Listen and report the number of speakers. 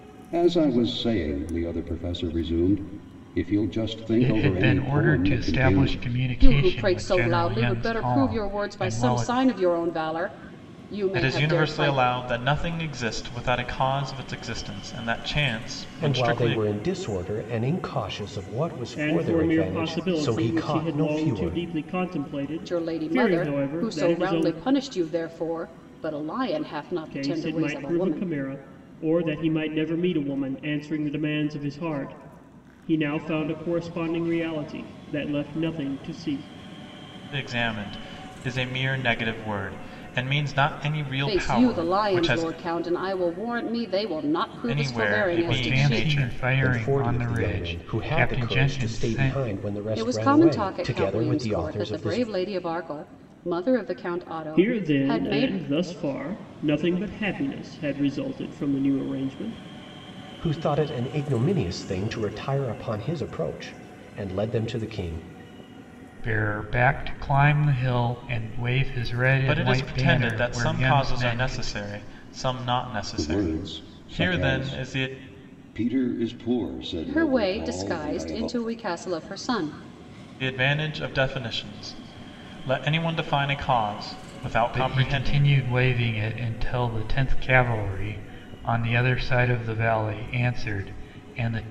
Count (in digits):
6